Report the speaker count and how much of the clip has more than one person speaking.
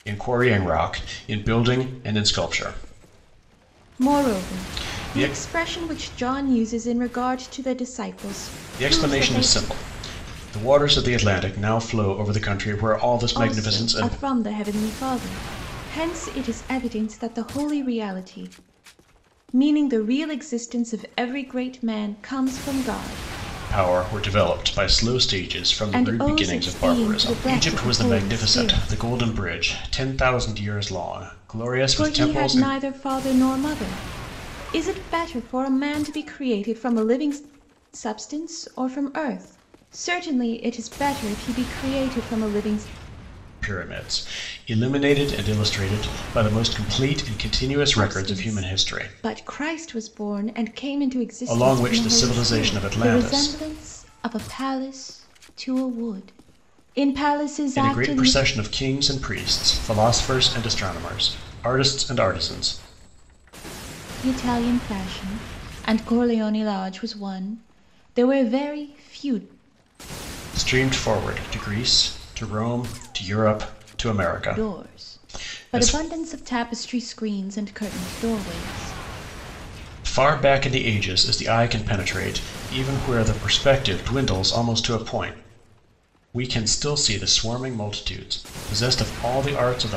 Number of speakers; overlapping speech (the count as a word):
two, about 14%